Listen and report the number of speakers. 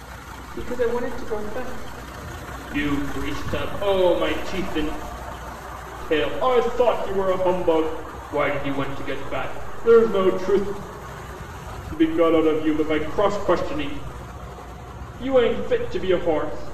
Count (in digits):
1